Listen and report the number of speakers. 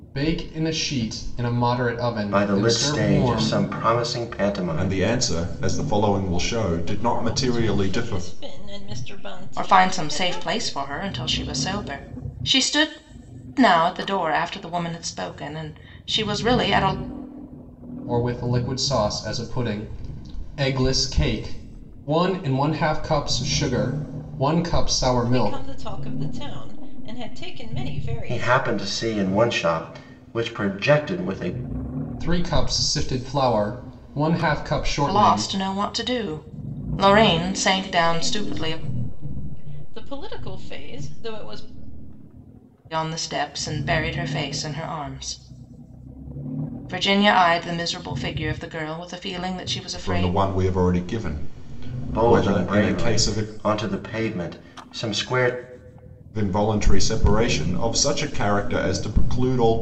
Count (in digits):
5